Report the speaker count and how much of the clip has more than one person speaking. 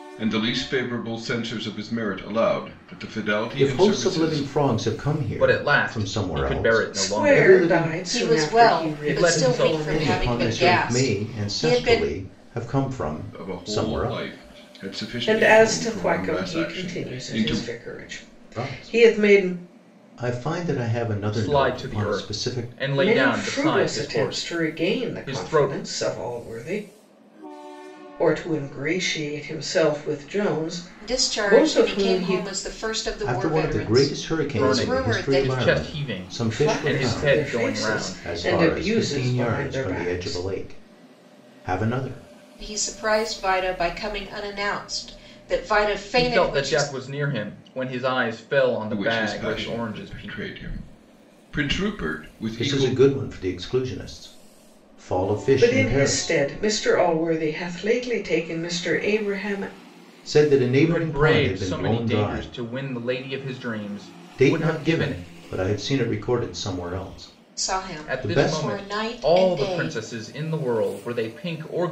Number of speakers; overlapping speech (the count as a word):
five, about 47%